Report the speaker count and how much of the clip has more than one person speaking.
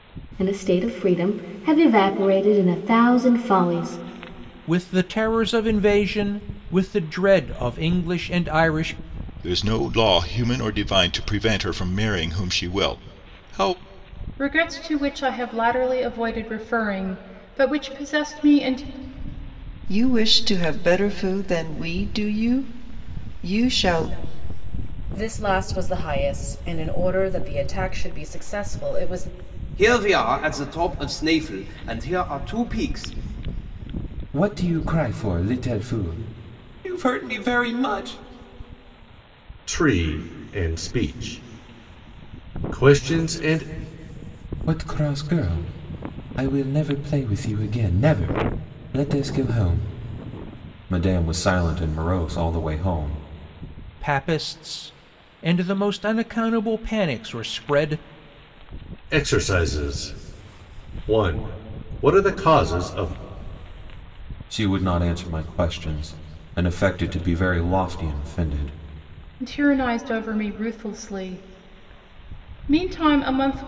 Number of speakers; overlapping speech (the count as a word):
nine, no overlap